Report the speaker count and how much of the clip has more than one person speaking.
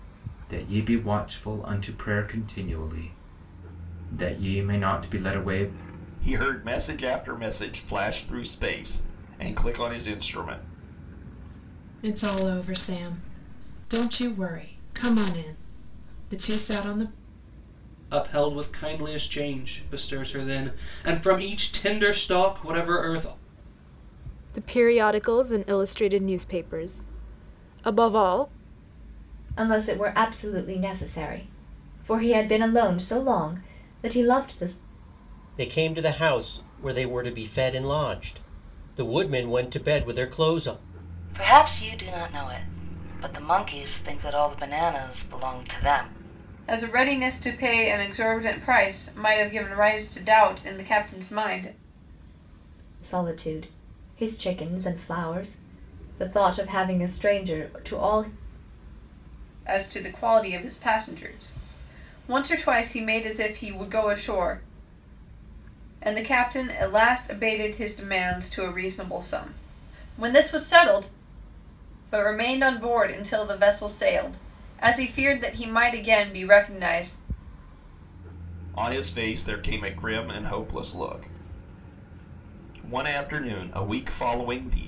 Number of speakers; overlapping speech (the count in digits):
9, no overlap